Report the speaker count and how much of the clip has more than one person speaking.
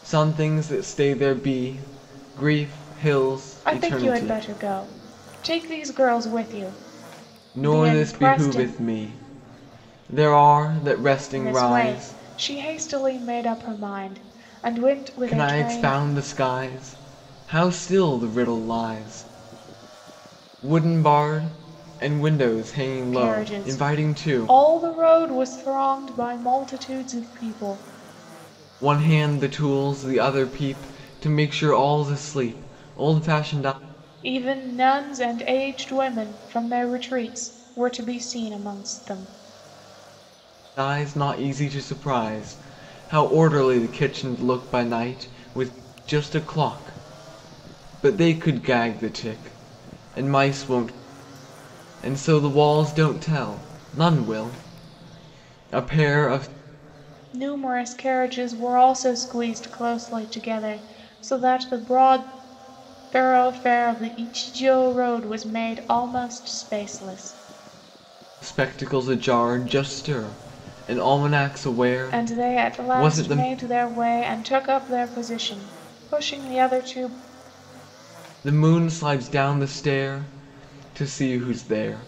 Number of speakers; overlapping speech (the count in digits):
2, about 8%